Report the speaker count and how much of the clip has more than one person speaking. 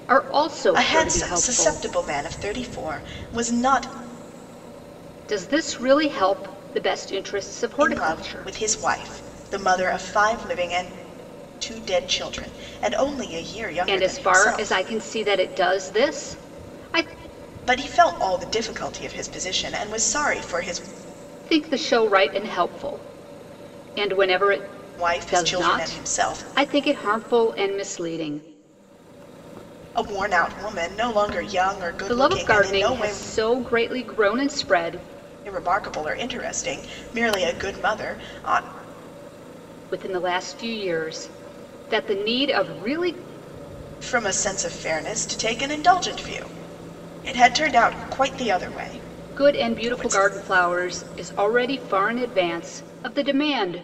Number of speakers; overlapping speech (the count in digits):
2, about 12%